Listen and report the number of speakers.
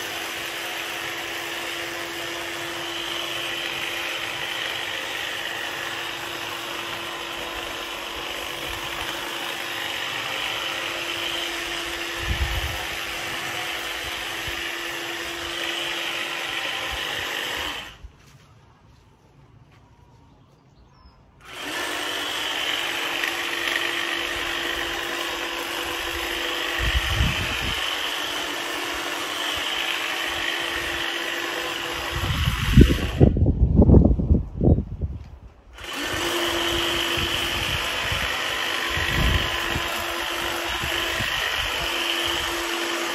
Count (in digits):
0